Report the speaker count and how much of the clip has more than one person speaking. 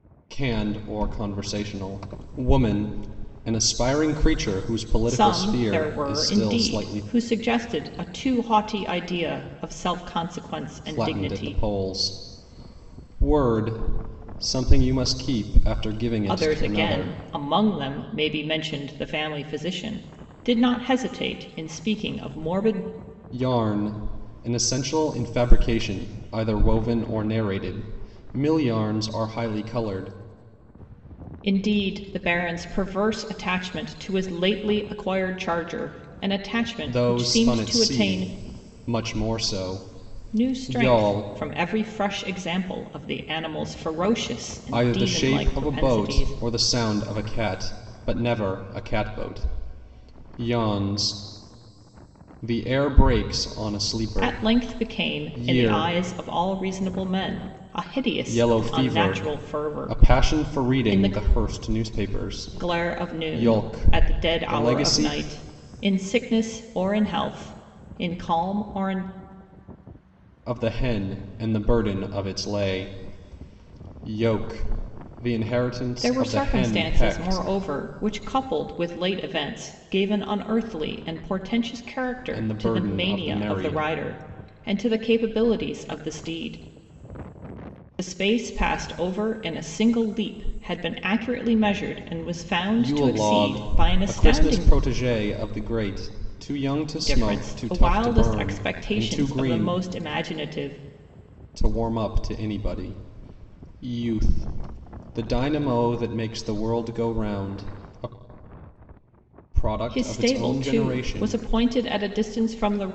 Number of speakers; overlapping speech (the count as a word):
two, about 21%